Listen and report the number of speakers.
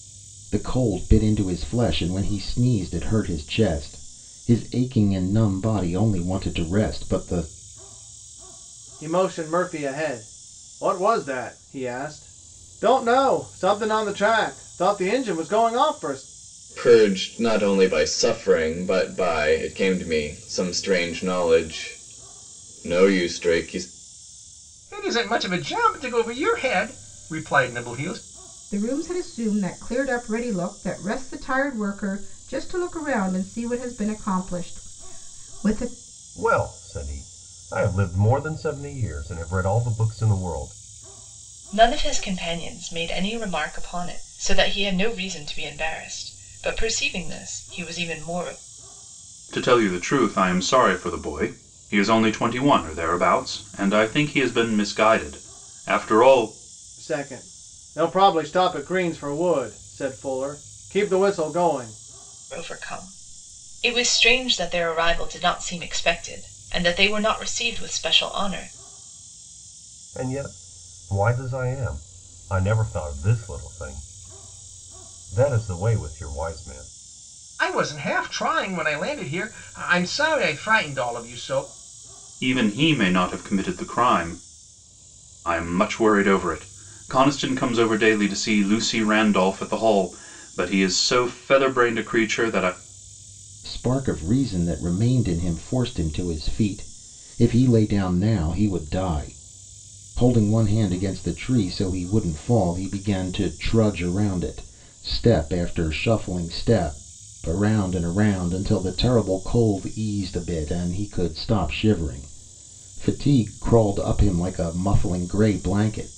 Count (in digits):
8